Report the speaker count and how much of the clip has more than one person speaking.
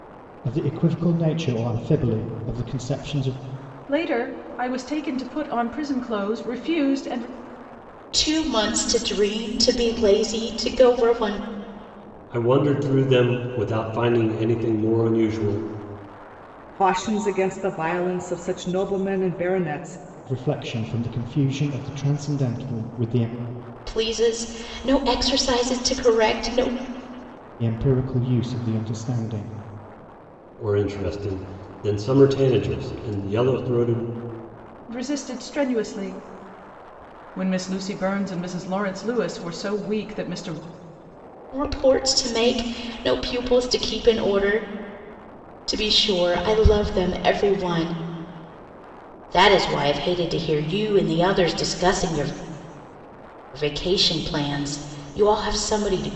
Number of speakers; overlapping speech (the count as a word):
five, no overlap